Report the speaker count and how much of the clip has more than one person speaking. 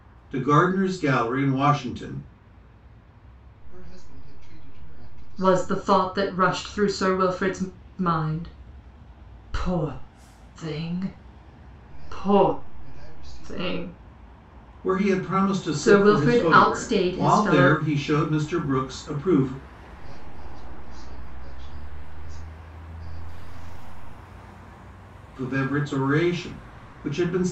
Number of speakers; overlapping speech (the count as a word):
three, about 13%